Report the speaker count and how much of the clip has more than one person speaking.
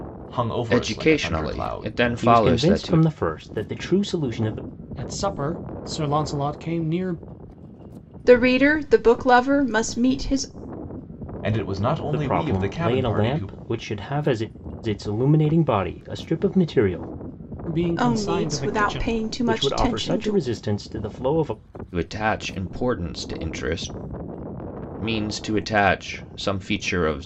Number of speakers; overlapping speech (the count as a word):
five, about 21%